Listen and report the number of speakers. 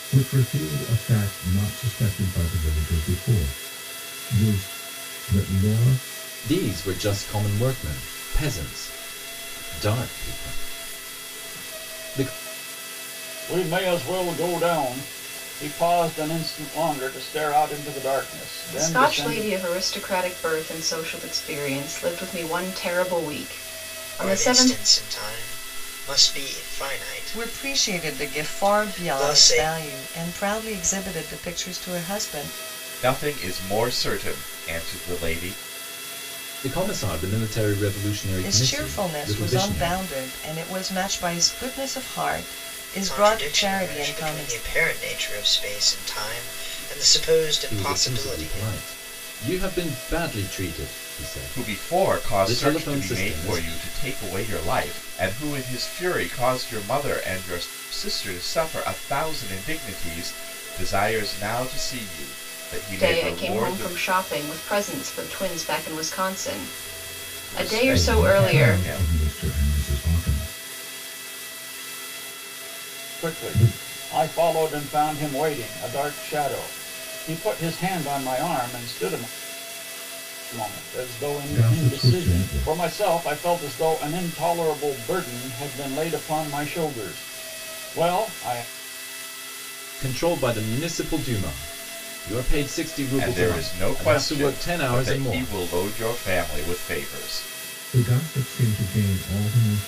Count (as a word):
seven